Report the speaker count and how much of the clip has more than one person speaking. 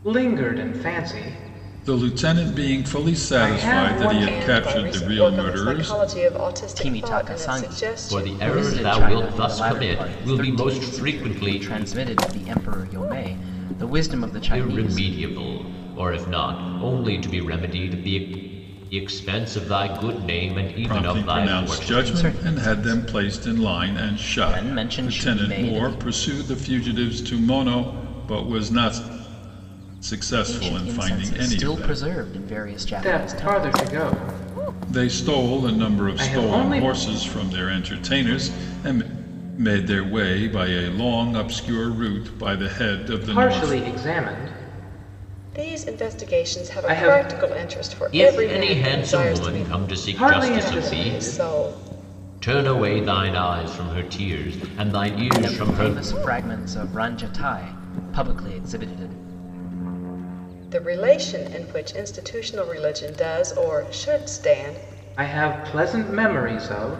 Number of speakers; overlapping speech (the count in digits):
5, about 38%